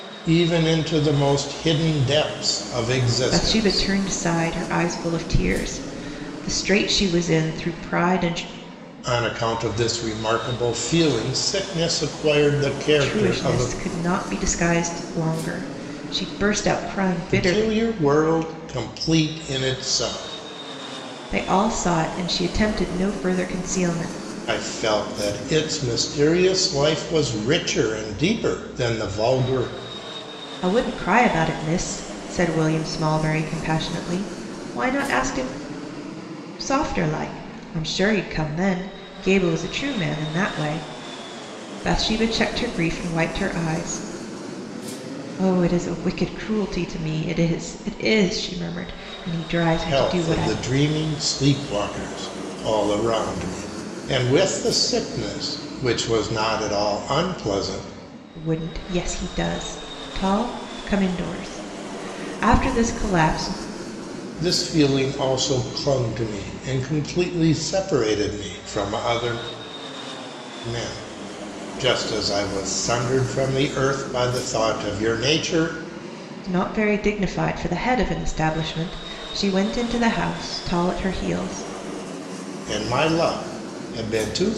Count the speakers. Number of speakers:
two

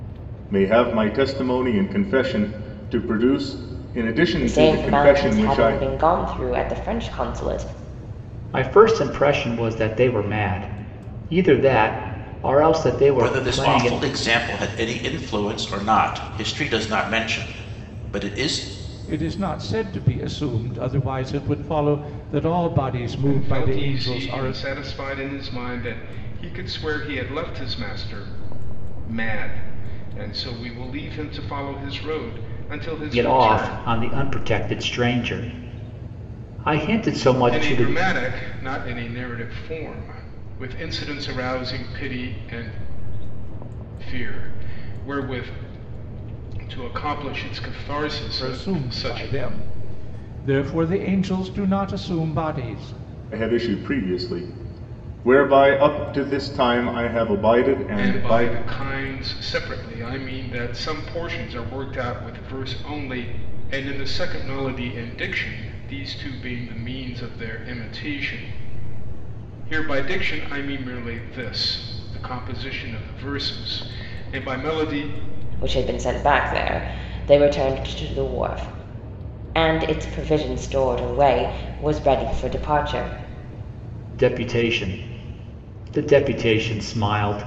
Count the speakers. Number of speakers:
six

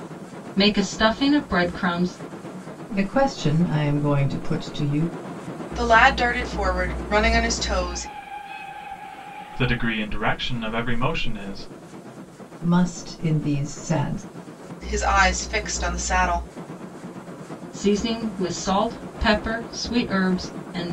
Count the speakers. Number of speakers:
four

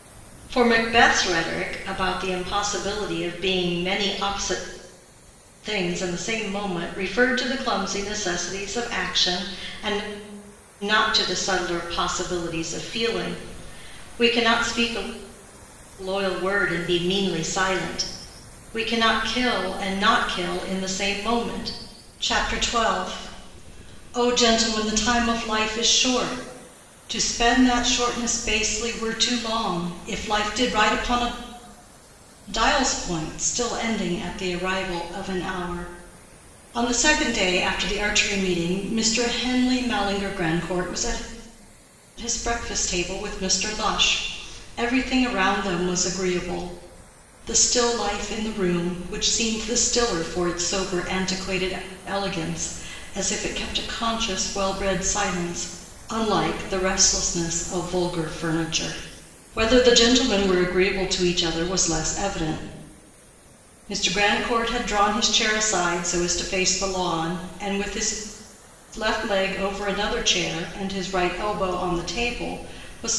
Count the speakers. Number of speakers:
one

